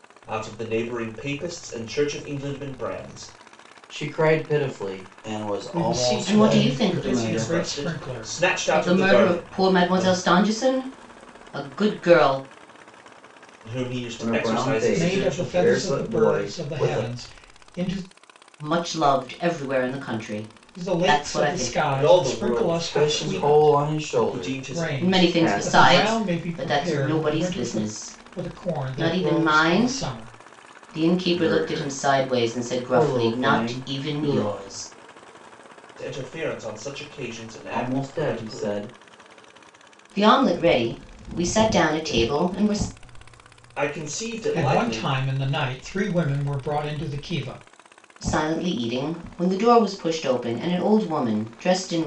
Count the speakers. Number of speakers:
4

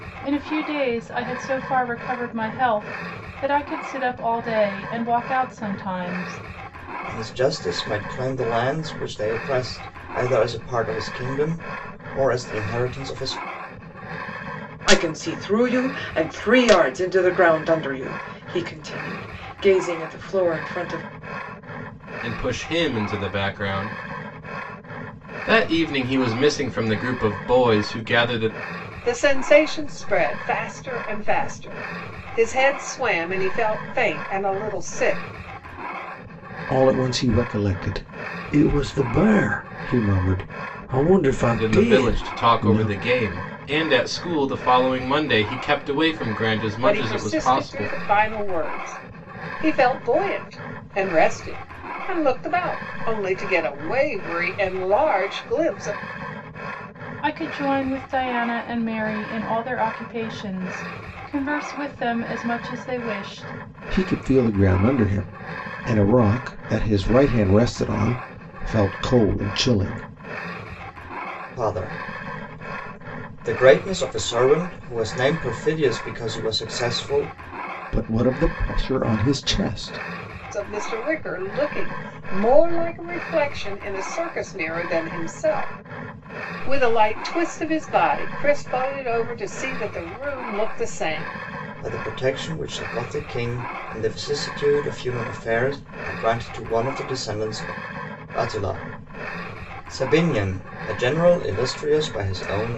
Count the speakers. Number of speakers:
6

